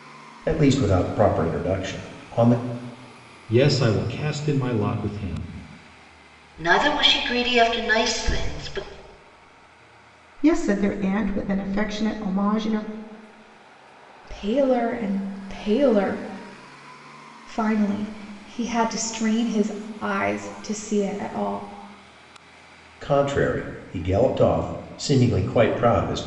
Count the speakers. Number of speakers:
five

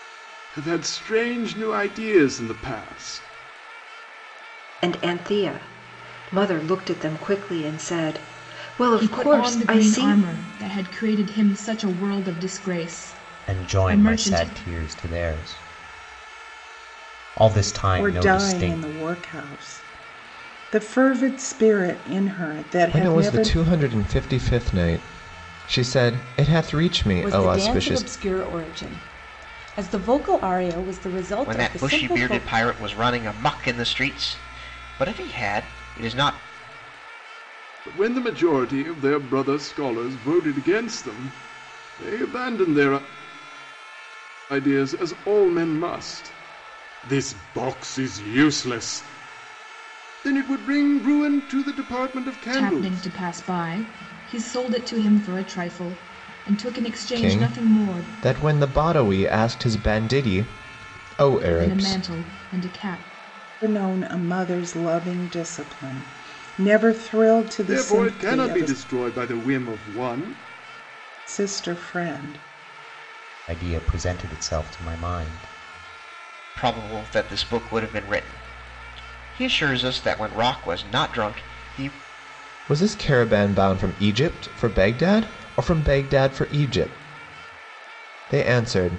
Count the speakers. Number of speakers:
eight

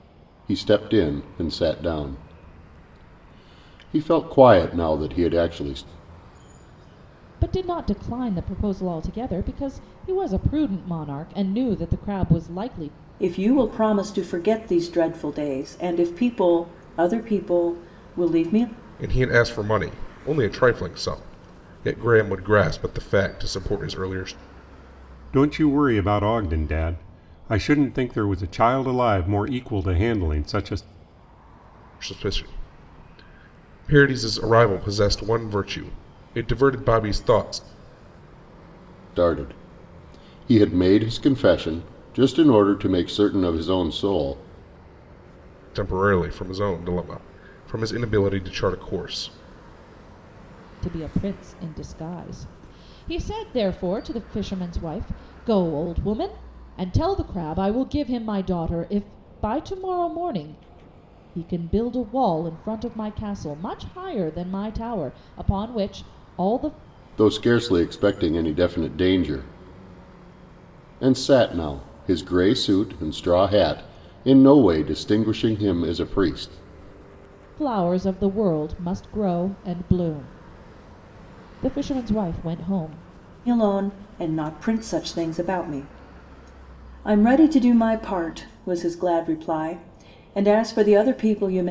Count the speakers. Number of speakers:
five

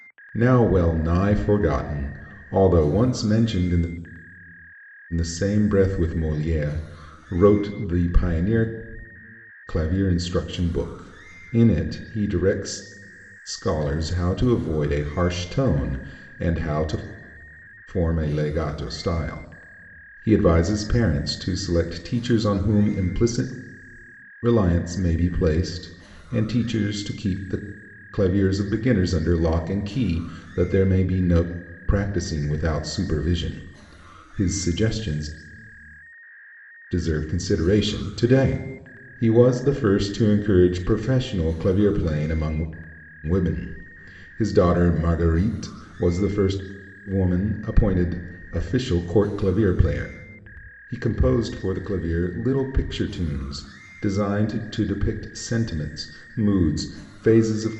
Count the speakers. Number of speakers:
one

